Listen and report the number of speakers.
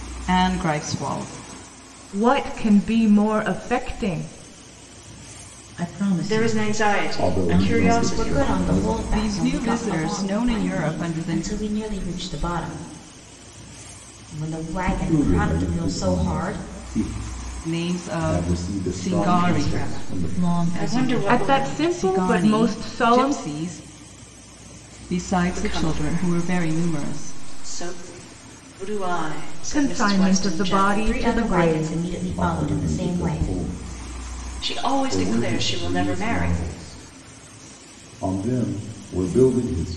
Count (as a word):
six